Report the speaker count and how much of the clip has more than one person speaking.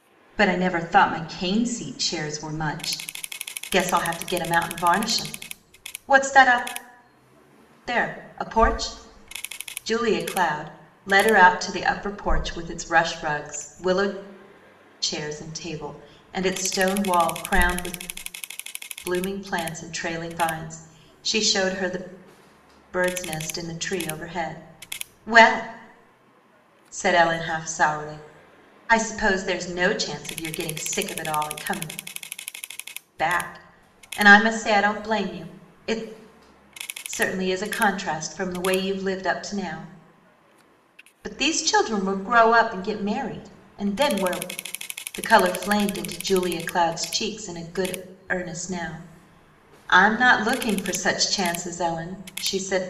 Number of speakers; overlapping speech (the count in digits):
1, no overlap